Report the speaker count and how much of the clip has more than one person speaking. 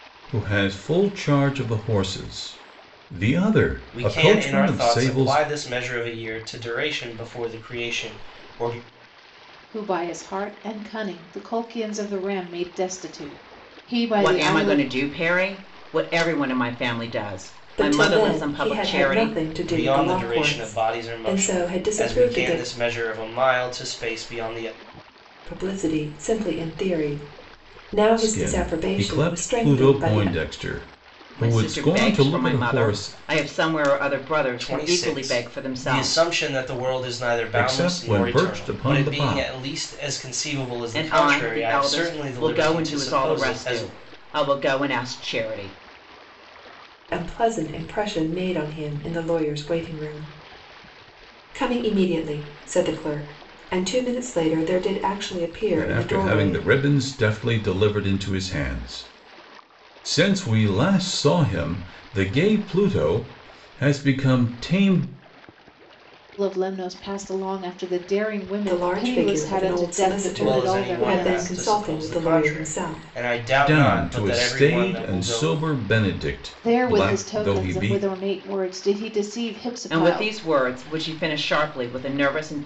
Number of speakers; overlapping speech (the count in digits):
5, about 32%